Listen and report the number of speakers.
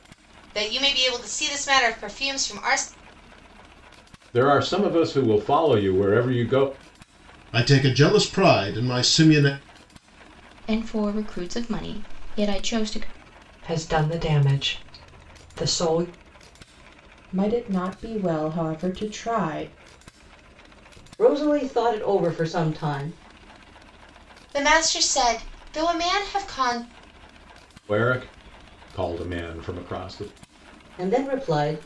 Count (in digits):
7